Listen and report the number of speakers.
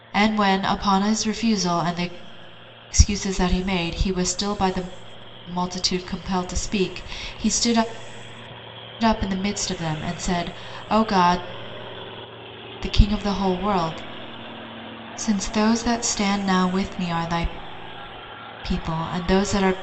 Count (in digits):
1